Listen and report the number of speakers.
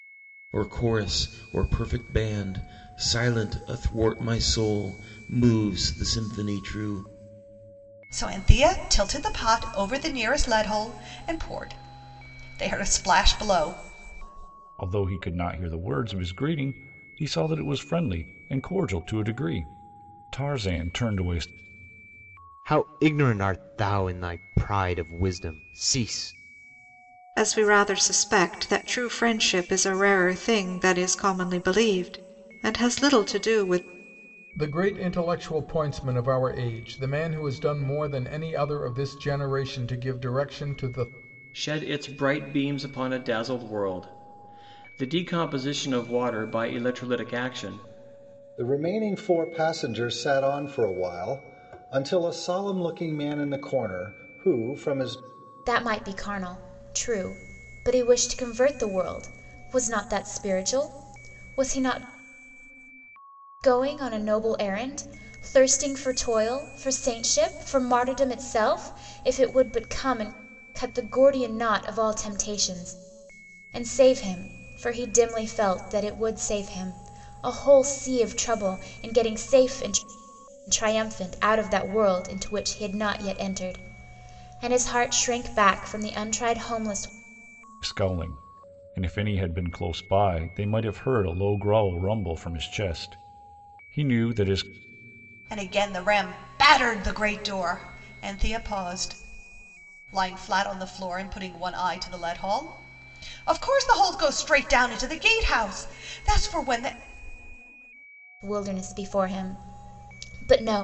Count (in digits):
9